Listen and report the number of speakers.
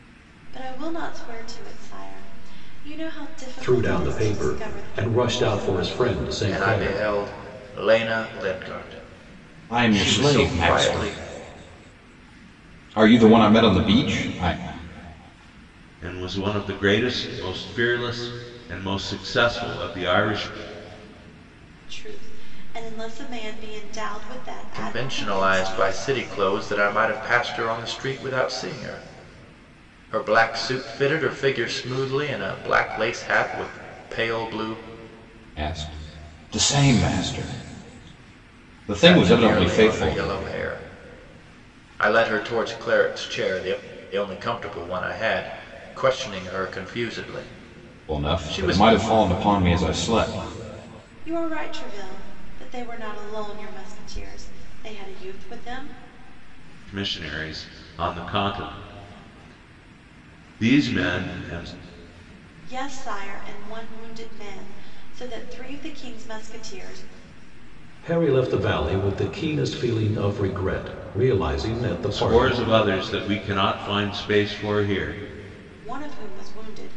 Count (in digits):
5